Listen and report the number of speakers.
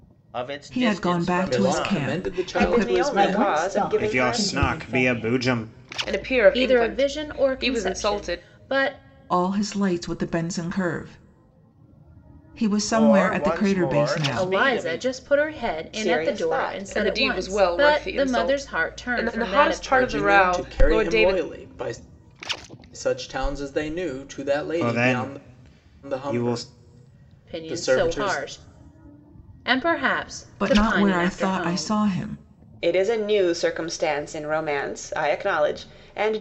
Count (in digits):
8